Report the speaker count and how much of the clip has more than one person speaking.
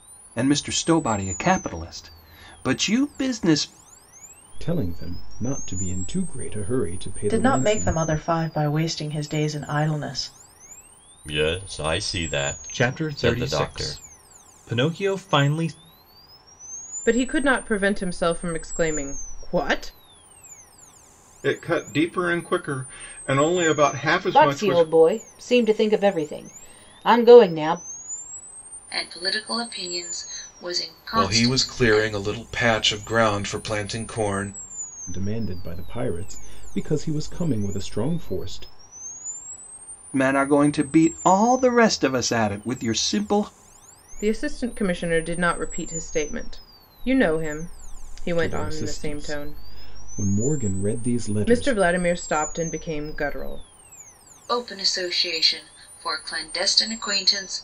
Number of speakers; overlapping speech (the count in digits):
10, about 9%